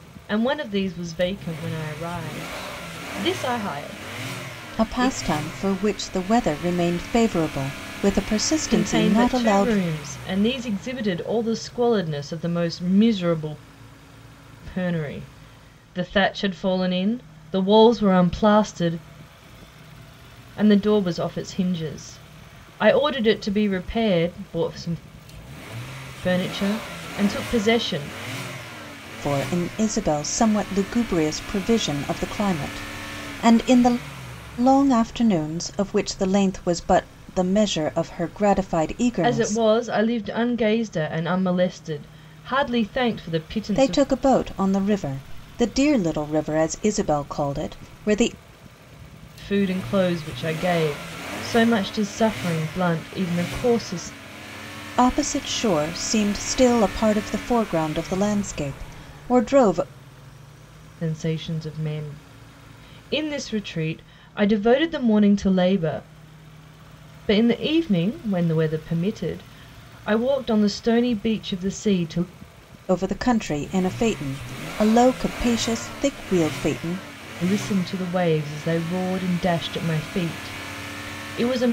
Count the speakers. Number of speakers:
2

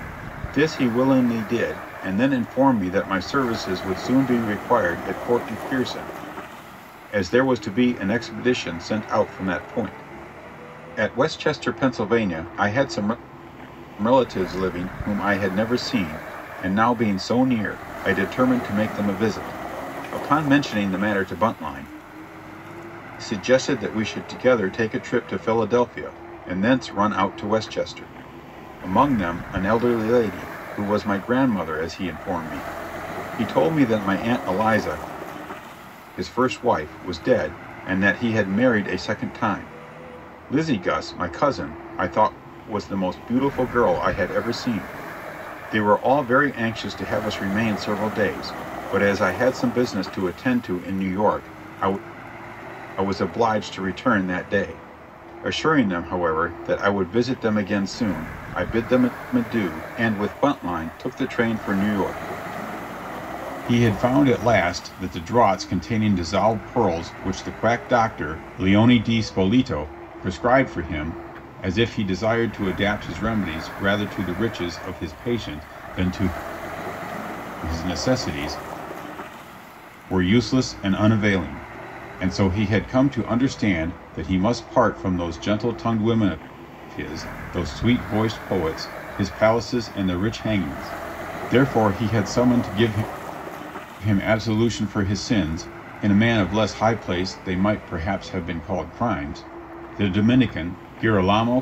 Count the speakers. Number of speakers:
1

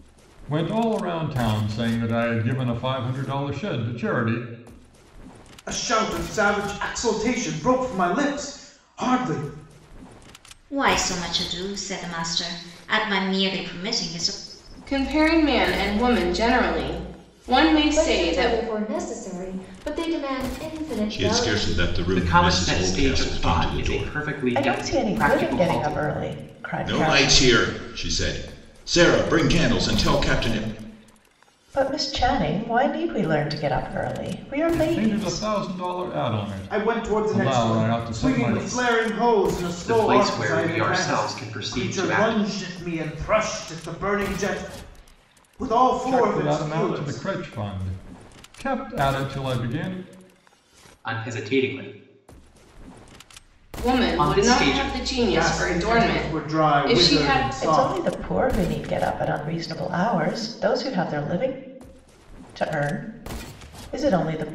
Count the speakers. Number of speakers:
8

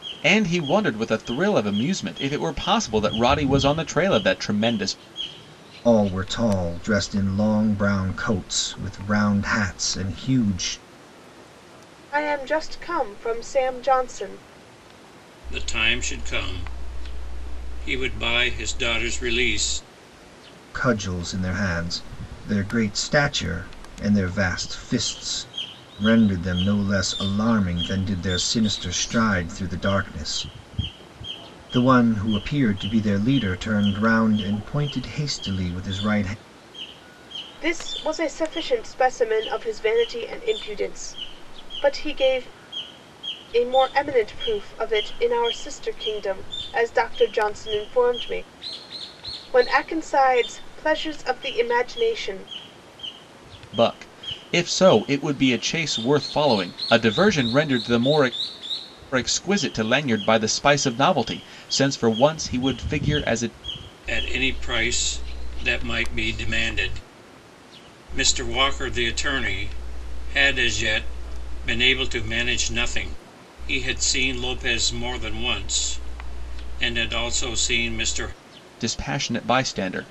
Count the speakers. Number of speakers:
4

